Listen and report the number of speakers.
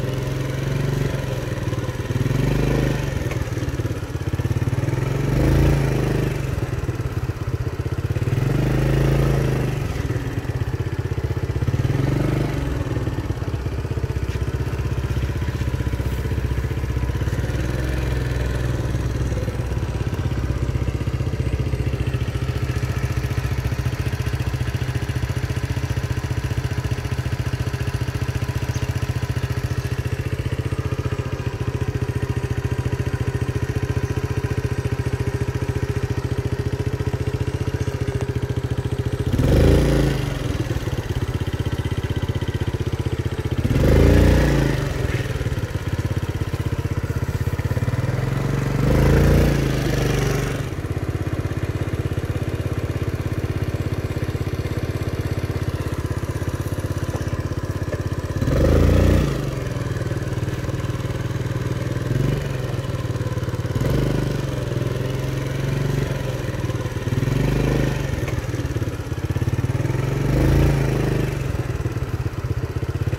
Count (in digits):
0